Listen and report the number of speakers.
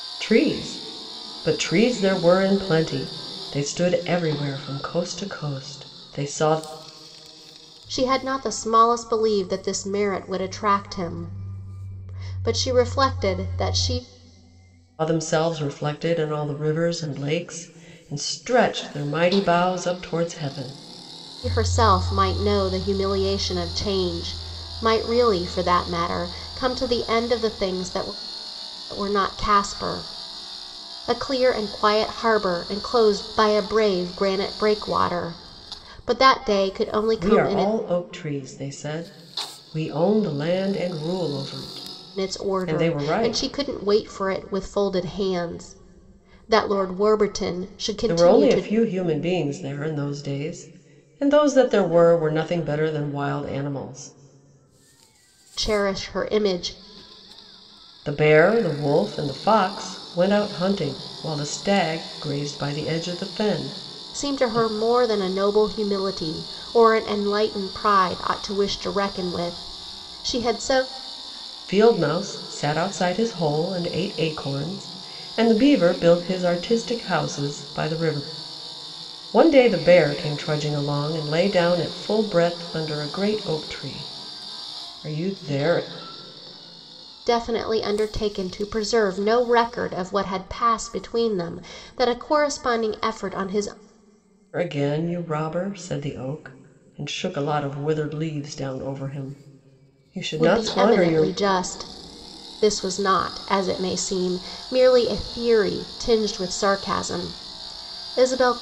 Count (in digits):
2